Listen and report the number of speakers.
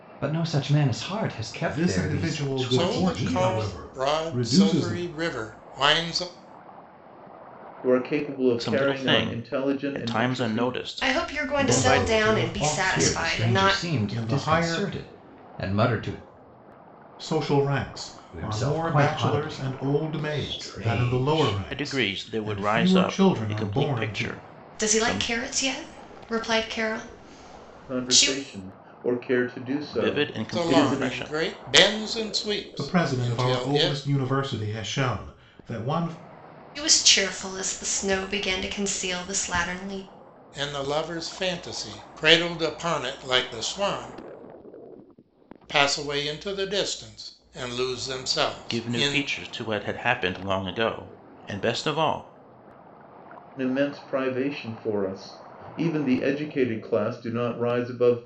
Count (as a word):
six